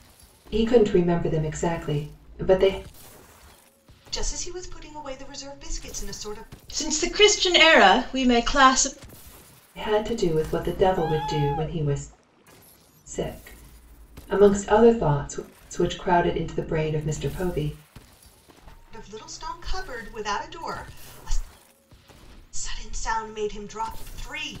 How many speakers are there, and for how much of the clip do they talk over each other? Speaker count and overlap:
3, no overlap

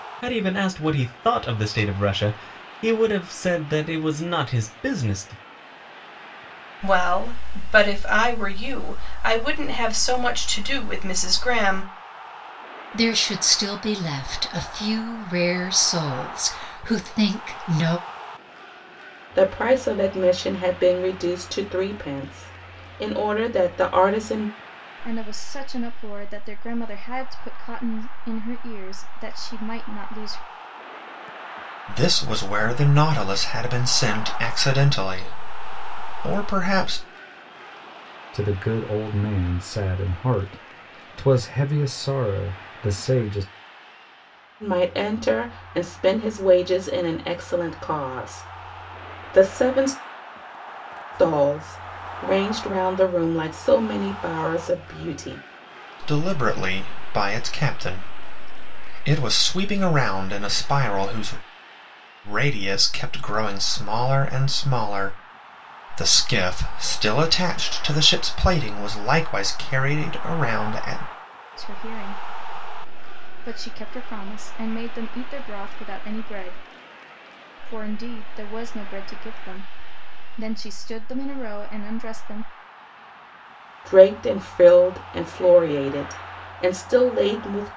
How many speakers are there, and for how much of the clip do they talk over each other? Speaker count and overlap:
7, no overlap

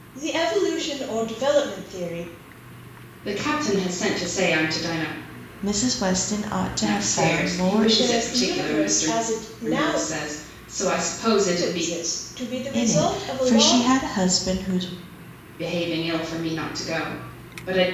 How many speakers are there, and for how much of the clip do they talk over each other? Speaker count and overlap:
3, about 23%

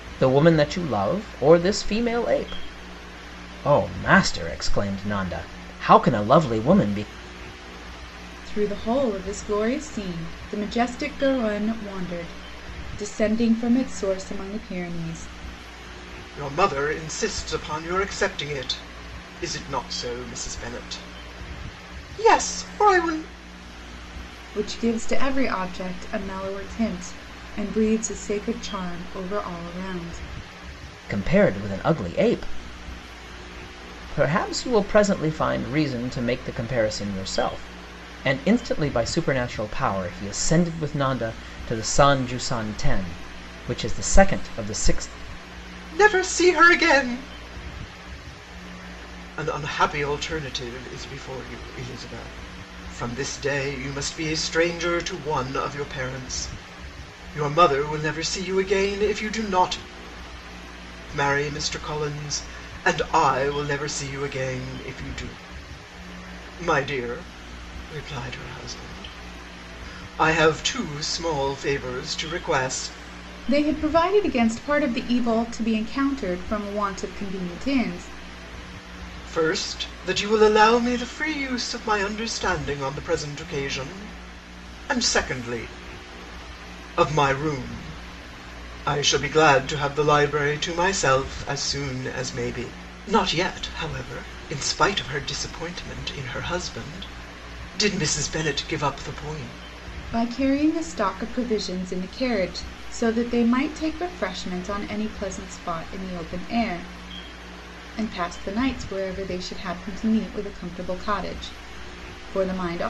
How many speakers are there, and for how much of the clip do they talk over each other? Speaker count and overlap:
3, no overlap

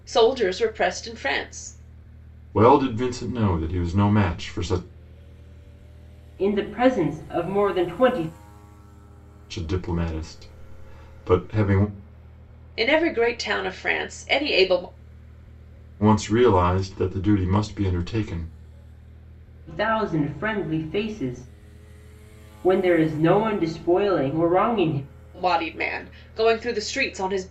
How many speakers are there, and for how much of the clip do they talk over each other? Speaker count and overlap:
3, no overlap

